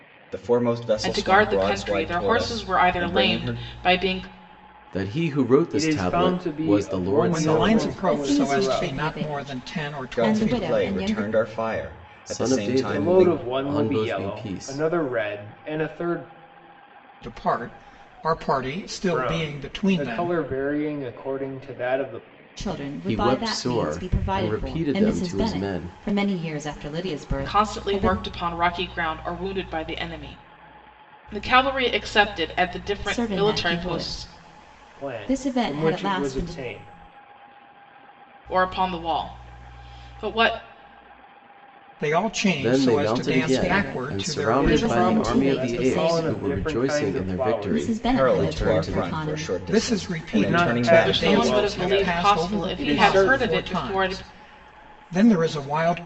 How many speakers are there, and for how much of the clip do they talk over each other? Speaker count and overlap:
six, about 54%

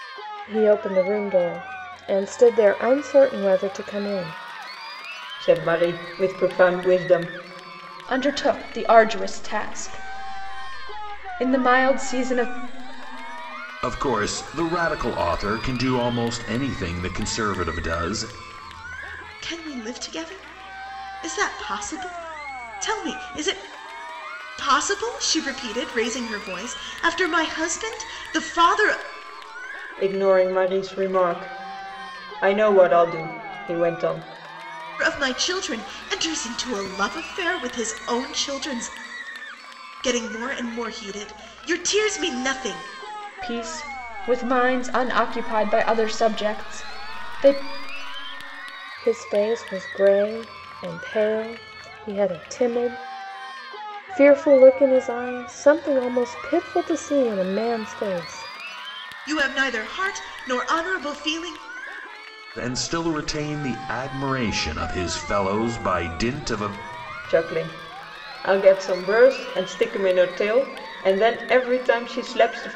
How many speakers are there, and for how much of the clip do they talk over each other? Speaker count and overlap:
five, no overlap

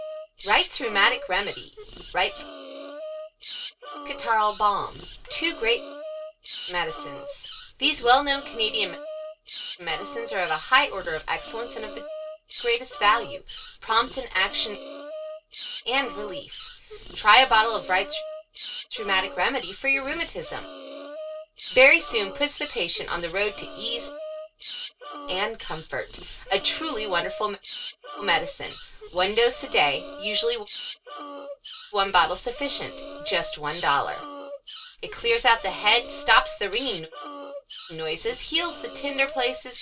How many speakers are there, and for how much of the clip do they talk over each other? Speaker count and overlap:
one, no overlap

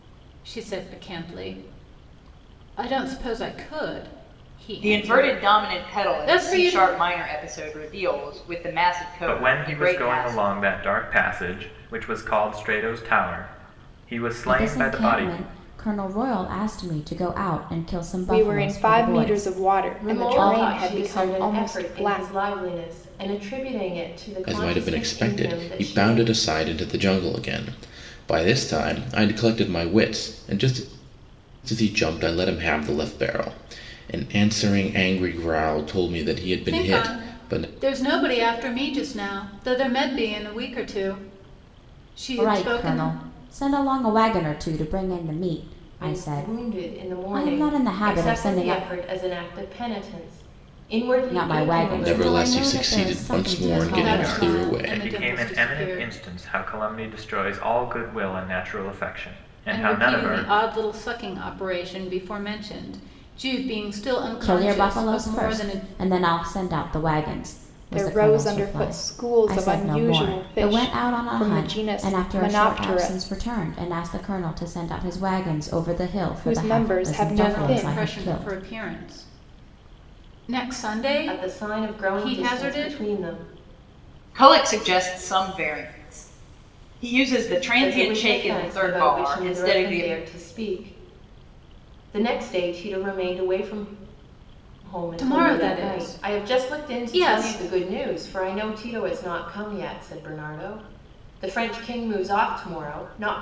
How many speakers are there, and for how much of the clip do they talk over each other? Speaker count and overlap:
seven, about 35%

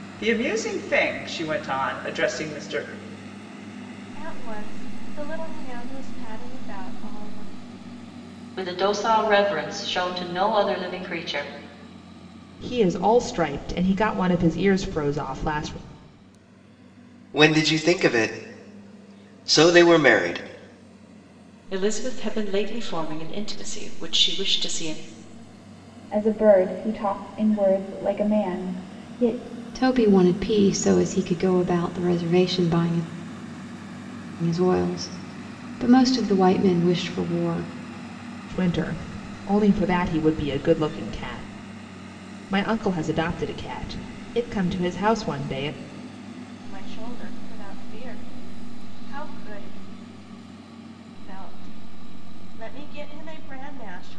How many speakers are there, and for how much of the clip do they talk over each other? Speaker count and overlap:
eight, no overlap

